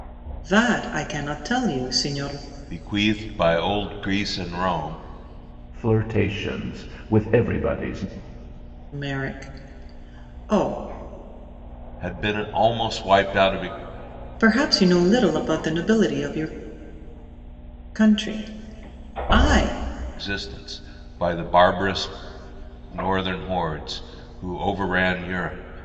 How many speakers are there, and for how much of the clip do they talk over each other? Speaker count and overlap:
3, no overlap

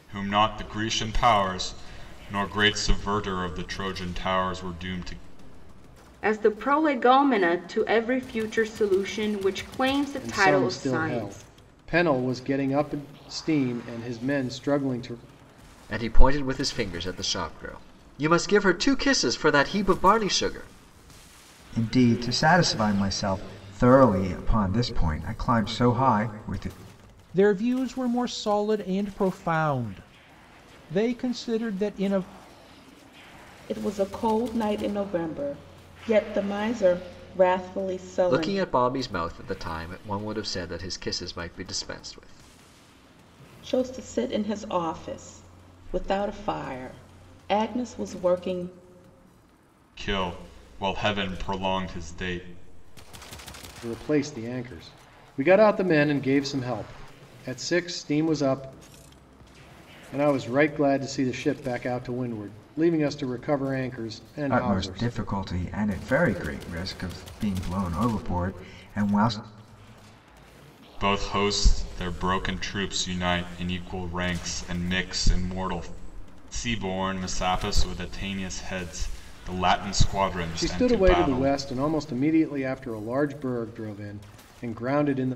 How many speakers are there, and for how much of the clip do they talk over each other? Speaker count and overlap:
7, about 4%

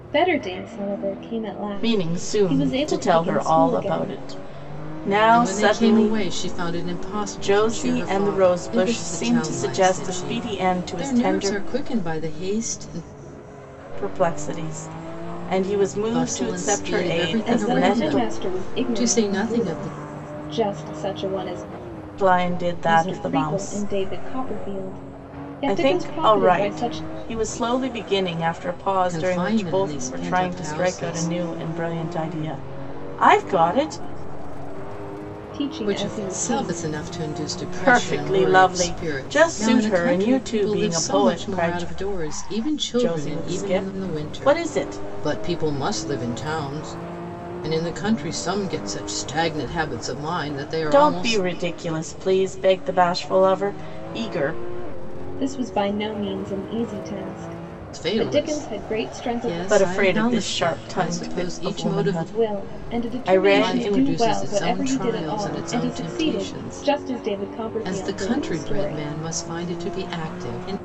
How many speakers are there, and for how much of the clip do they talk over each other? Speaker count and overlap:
3, about 49%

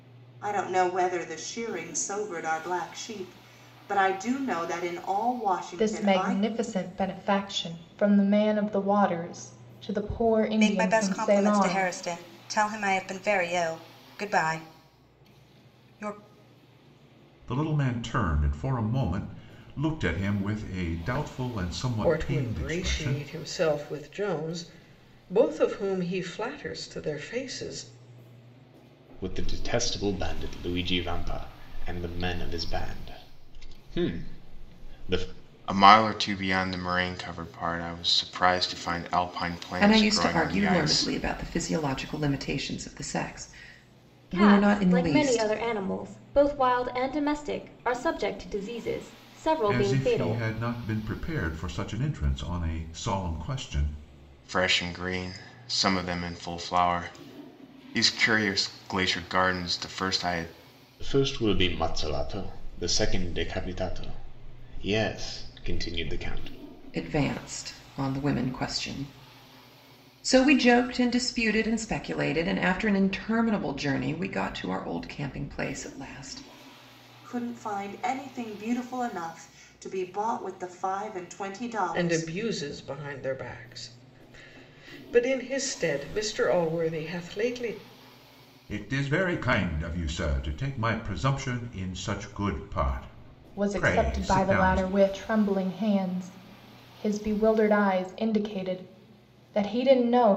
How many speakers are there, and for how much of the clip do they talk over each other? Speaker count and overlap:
9, about 8%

